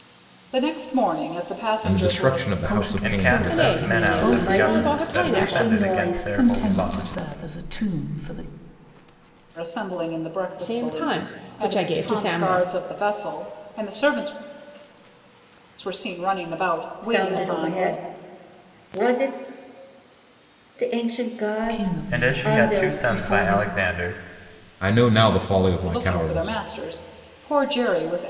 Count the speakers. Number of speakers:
6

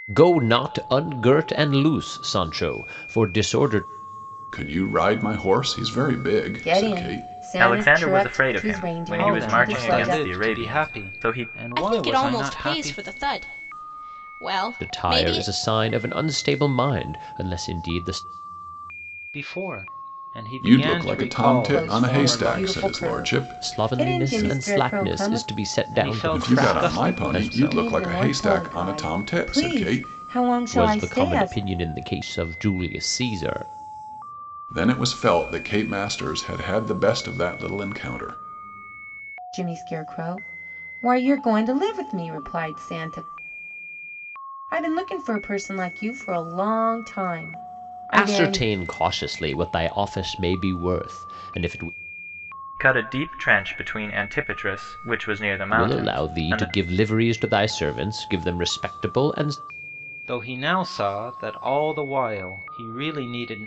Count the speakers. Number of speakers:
6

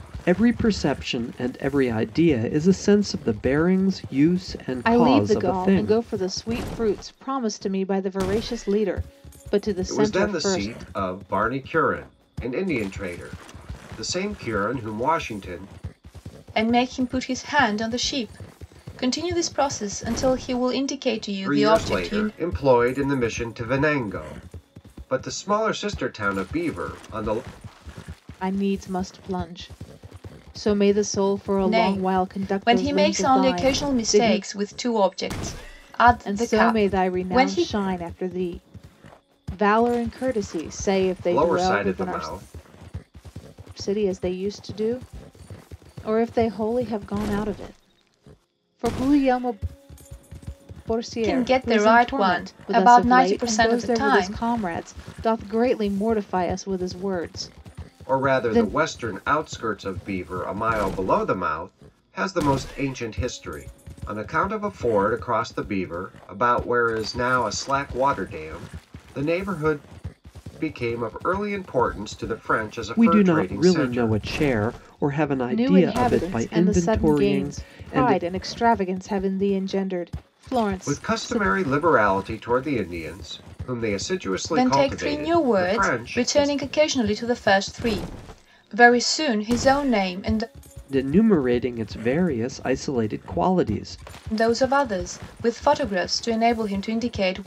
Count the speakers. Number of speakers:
4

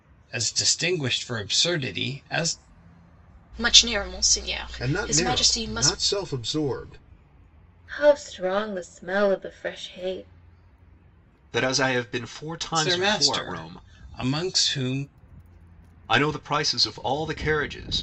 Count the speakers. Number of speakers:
5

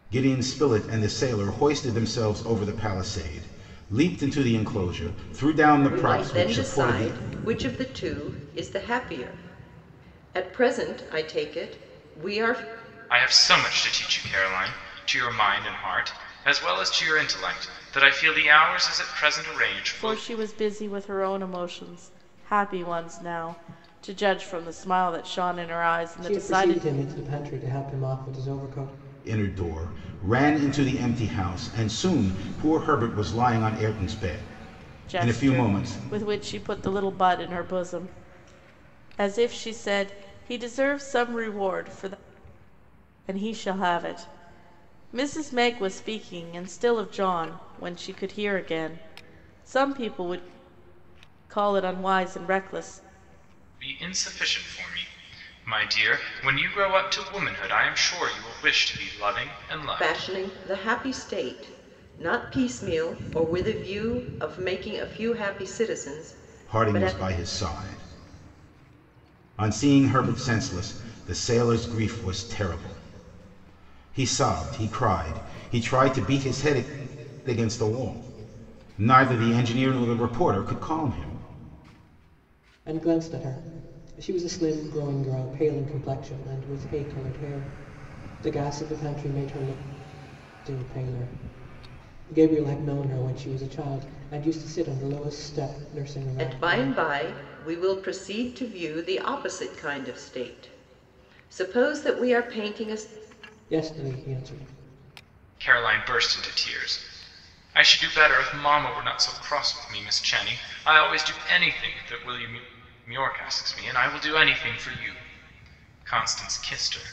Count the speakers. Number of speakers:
5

